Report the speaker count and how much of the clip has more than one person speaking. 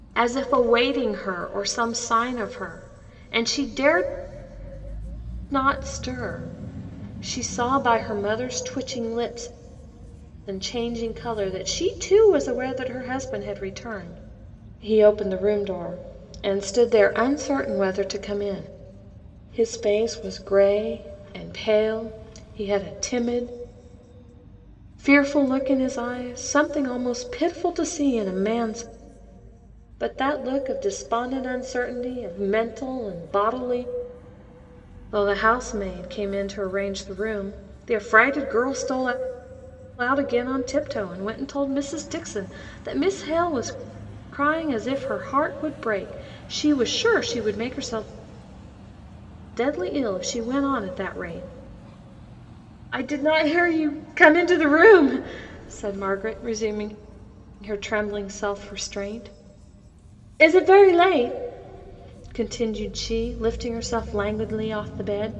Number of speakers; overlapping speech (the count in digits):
1, no overlap